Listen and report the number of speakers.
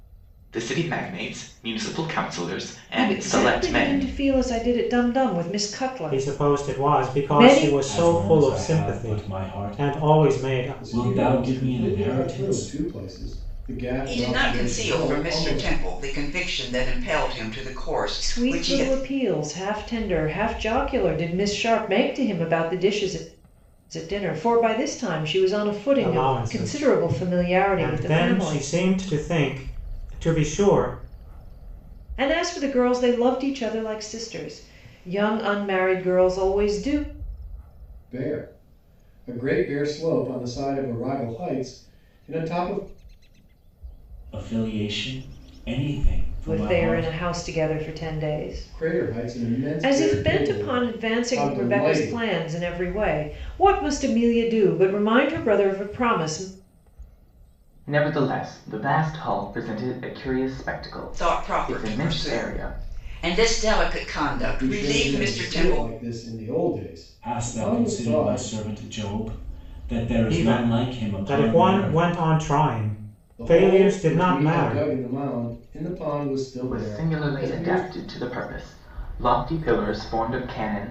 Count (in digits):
6